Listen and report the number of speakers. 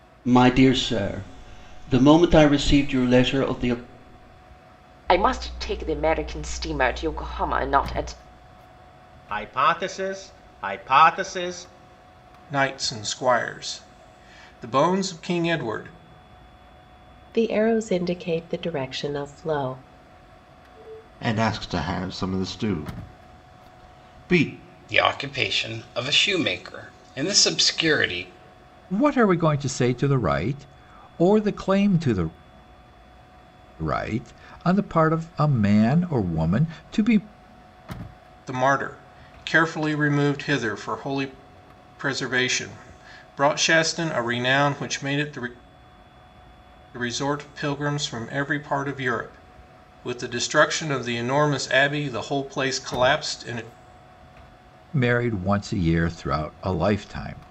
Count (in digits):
8